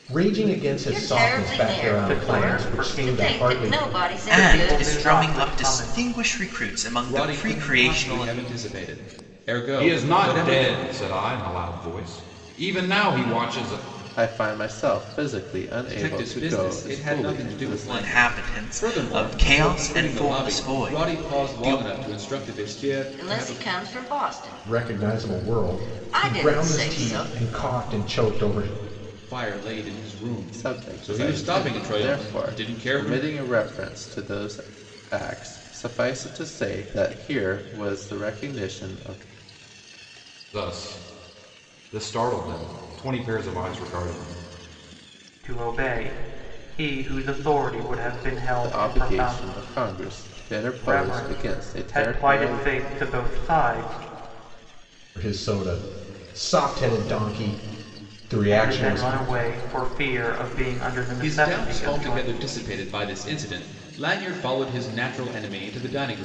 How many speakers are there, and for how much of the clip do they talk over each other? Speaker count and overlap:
7, about 36%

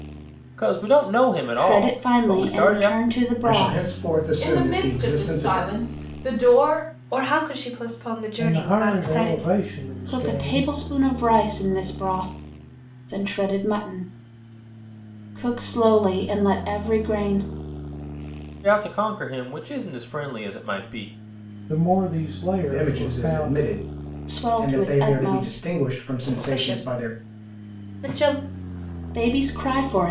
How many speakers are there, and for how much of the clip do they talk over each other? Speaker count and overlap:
6, about 28%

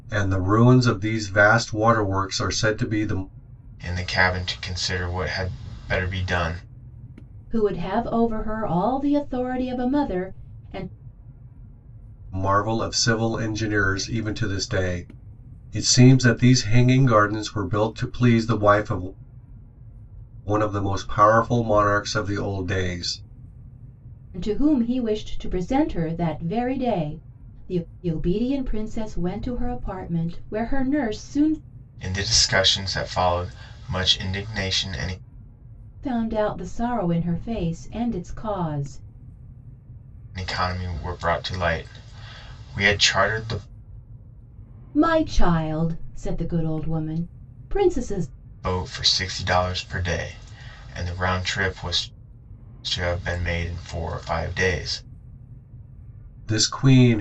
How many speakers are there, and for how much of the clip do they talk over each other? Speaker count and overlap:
3, no overlap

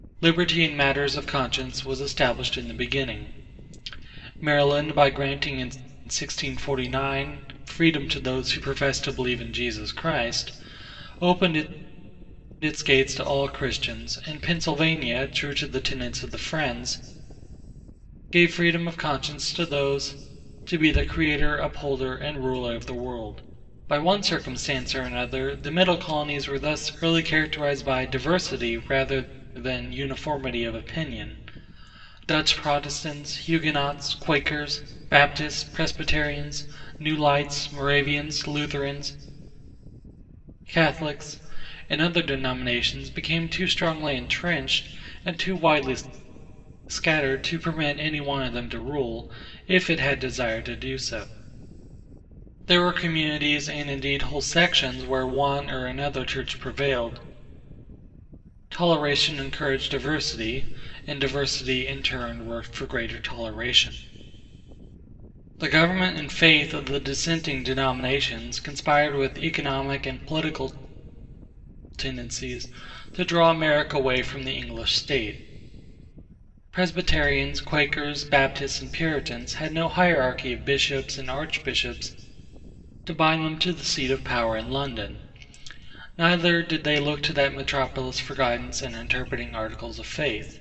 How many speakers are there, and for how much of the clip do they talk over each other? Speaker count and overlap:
1, no overlap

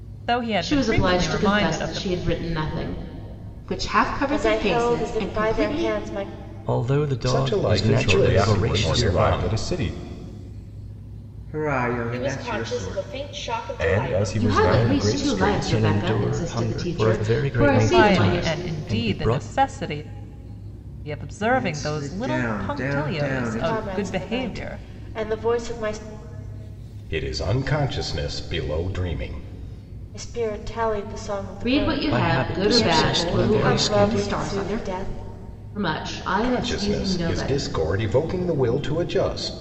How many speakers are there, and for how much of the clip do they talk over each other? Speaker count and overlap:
9, about 52%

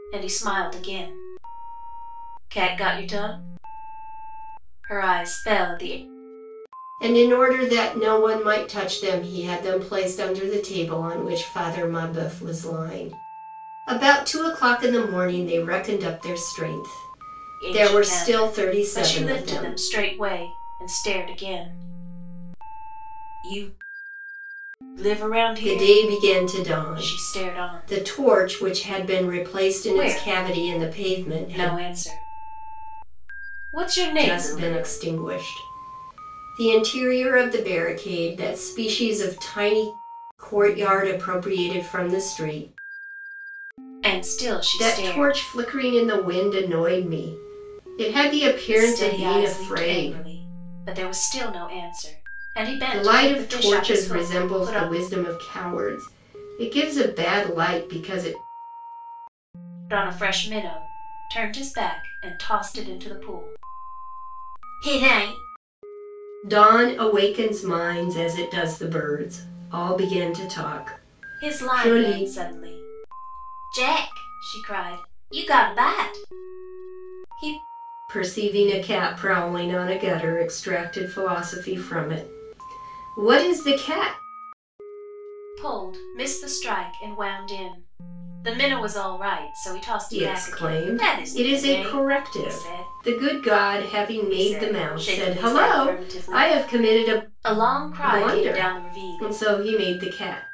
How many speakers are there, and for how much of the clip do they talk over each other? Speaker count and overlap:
2, about 19%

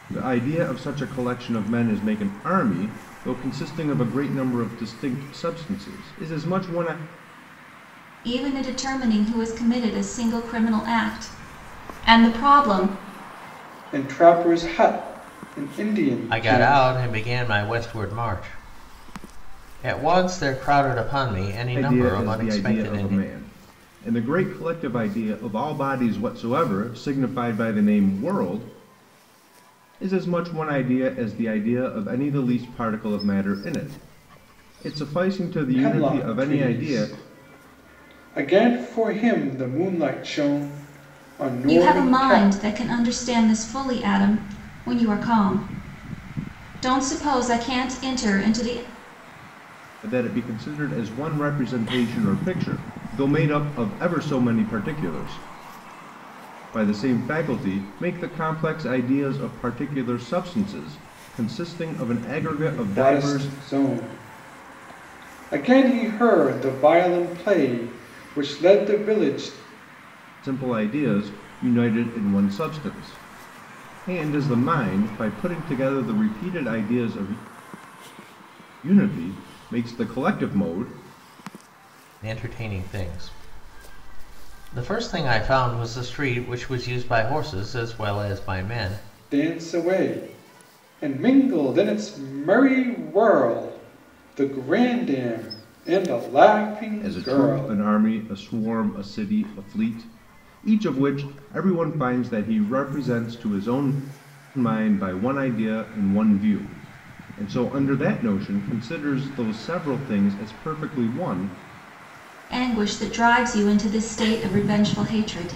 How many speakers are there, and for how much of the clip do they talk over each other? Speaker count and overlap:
4, about 5%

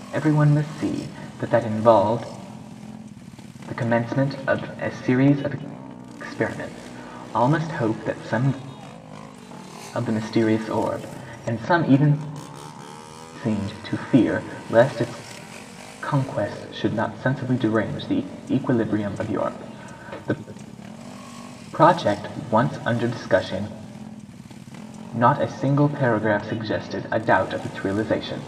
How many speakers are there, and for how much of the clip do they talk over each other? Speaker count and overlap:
1, no overlap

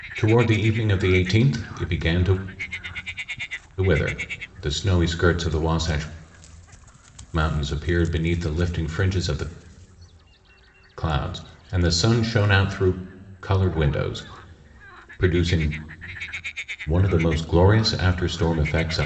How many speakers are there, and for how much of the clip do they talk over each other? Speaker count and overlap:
1, no overlap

